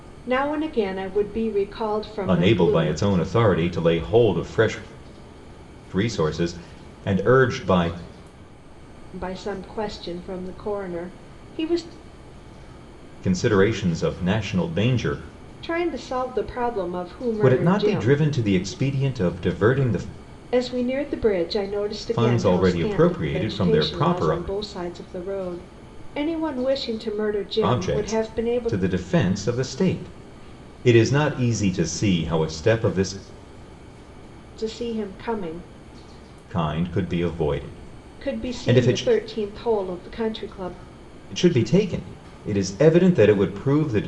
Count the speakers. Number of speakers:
two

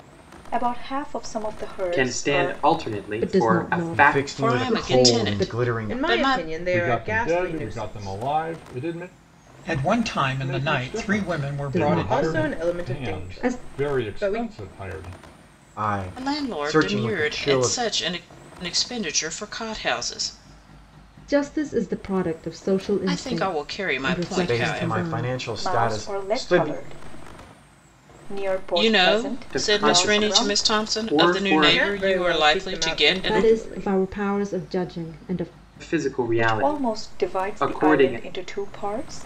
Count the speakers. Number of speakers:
eight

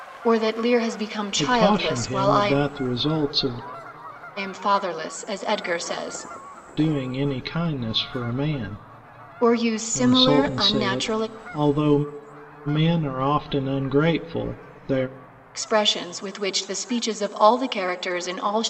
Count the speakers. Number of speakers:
two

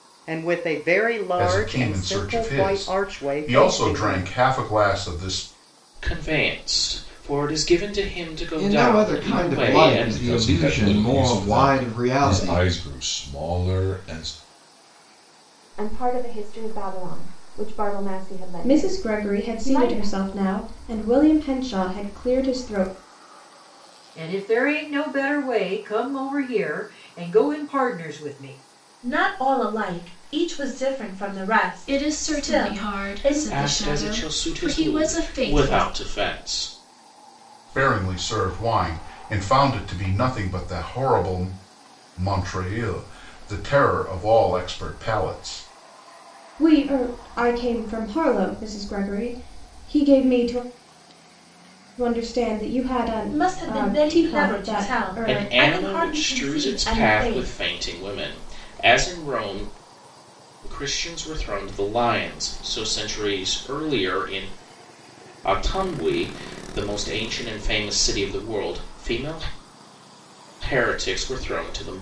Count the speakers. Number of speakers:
ten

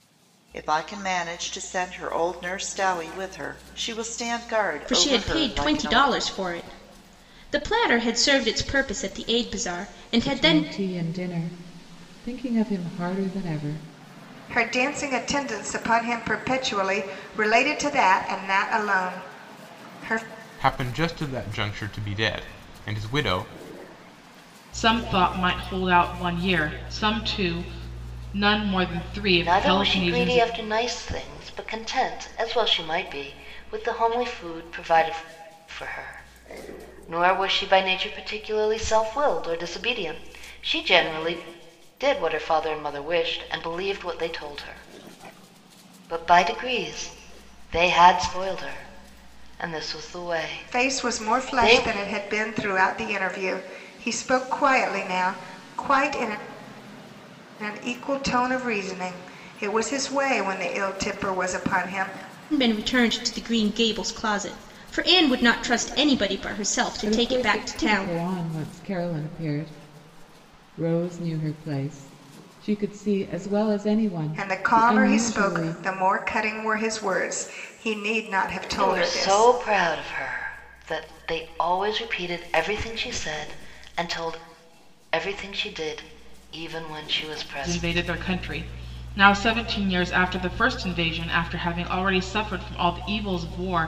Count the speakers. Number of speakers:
seven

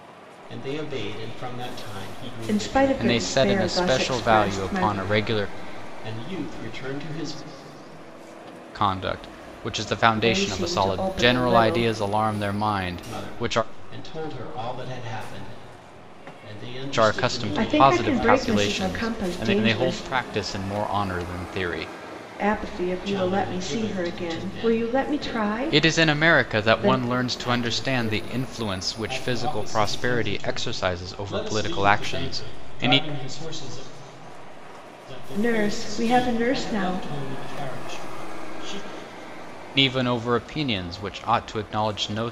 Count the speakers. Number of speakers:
three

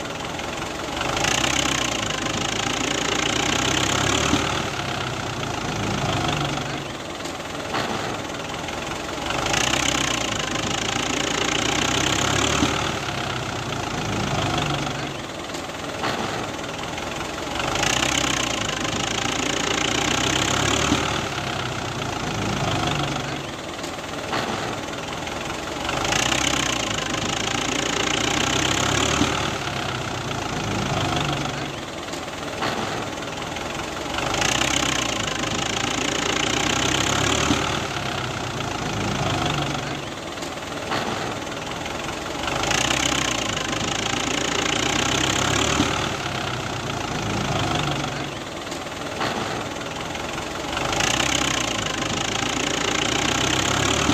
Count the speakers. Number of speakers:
zero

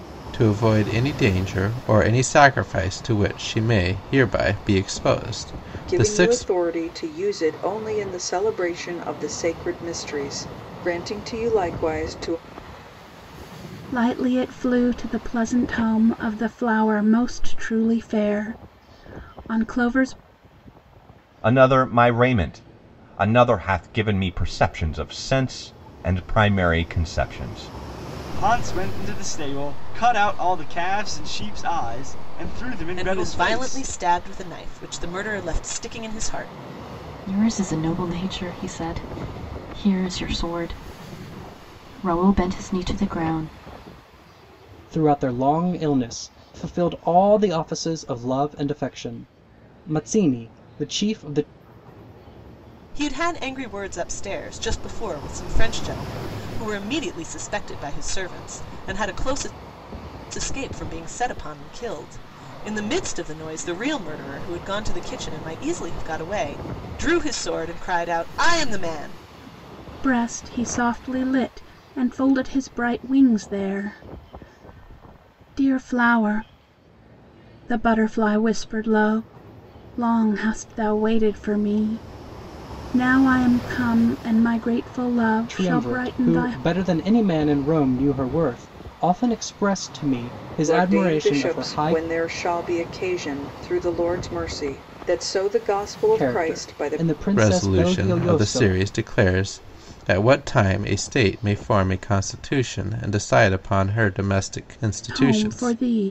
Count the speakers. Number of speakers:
eight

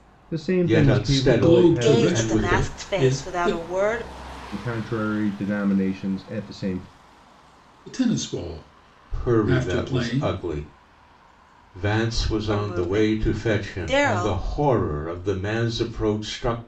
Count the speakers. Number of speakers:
four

